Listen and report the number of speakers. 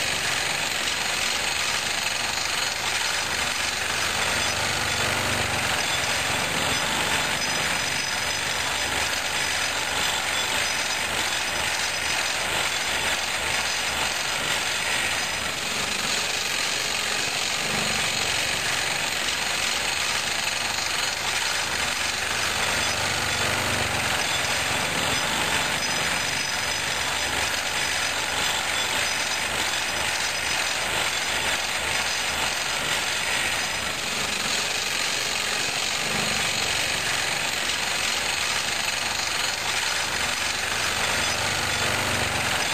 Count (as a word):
zero